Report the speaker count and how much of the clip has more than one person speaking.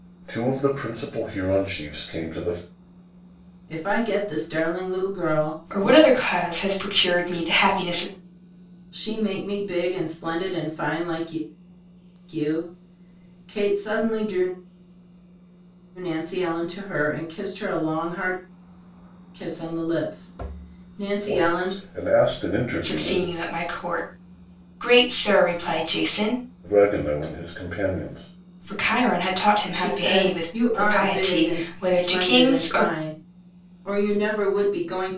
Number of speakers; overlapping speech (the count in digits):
3, about 13%